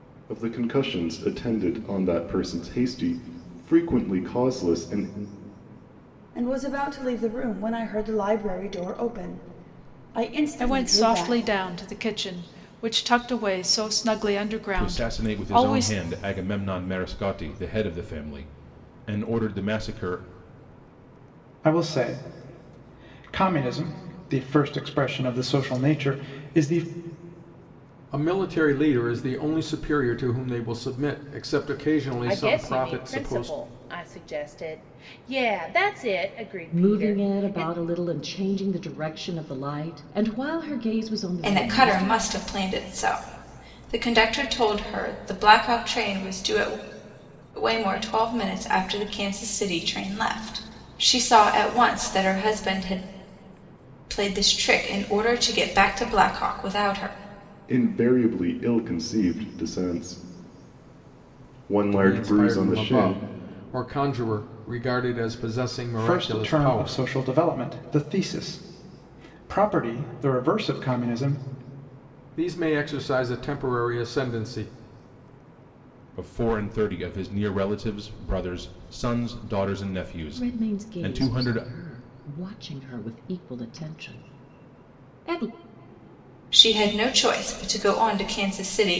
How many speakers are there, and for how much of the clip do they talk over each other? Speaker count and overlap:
9, about 10%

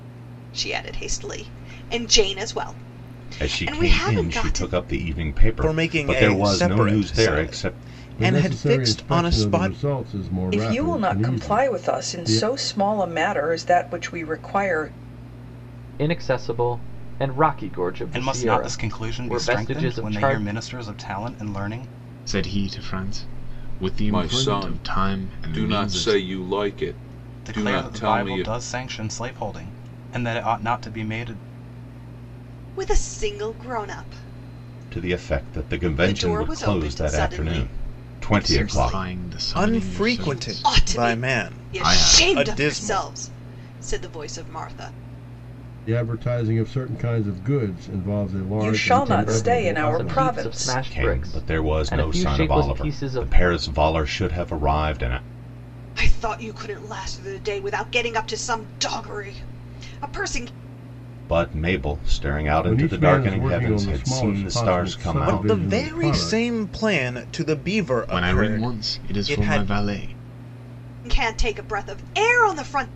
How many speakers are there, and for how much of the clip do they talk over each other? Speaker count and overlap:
9, about 44%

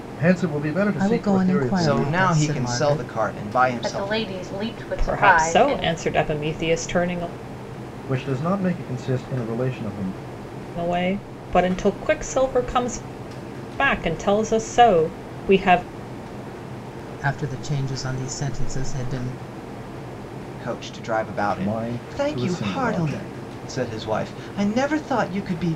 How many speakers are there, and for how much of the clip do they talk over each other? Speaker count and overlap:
5, about 21%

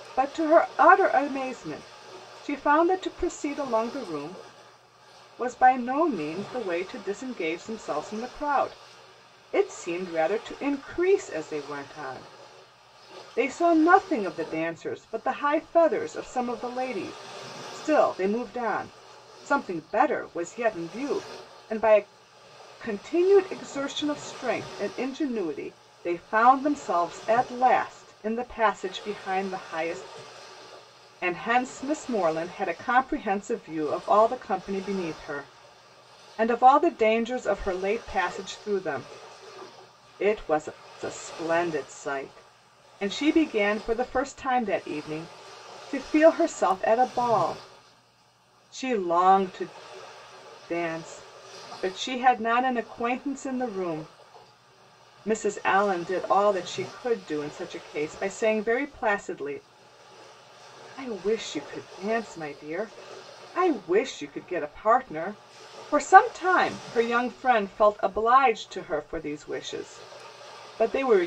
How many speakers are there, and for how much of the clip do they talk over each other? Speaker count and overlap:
1, no overlap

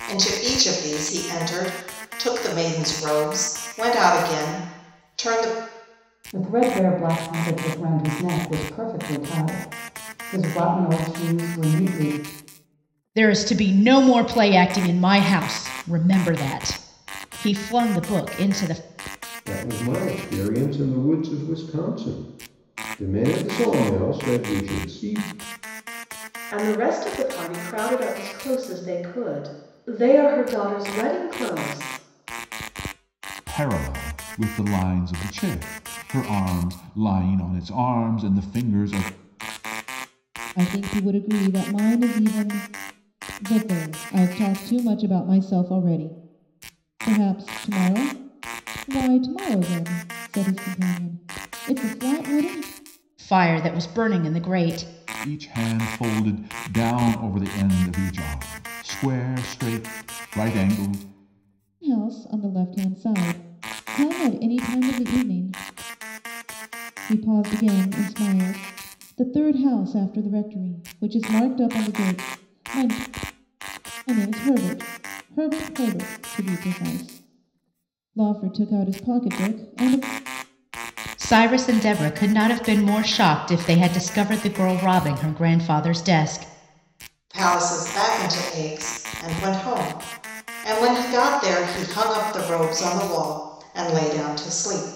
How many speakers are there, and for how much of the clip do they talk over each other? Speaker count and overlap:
7, no overlap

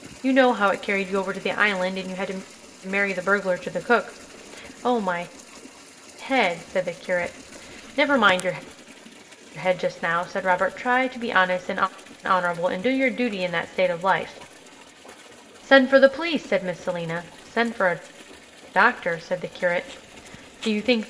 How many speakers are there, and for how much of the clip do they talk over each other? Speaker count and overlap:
1, no overlap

